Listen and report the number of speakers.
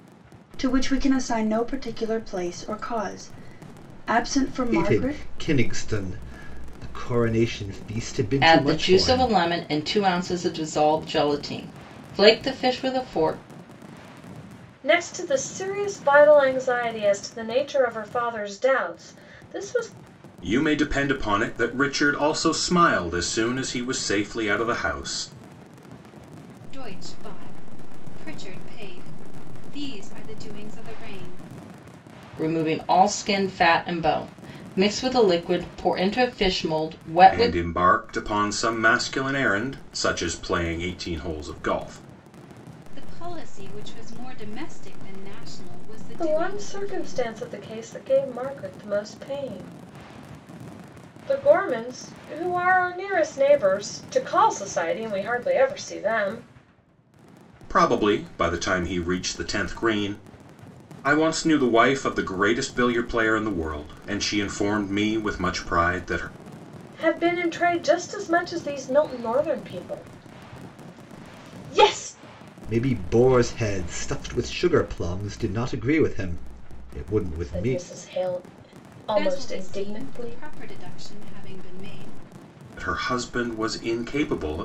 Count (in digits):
6